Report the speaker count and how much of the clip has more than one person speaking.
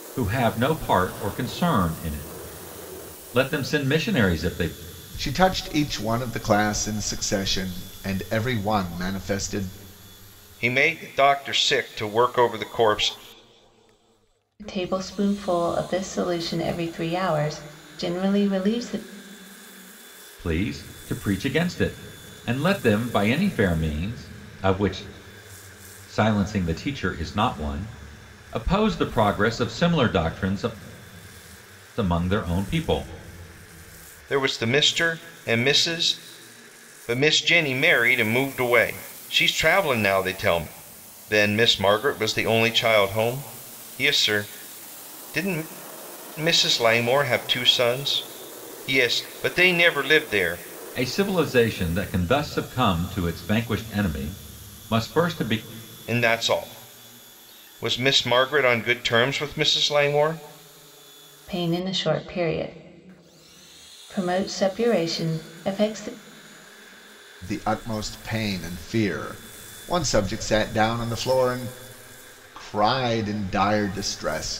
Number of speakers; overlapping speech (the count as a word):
four, no overlap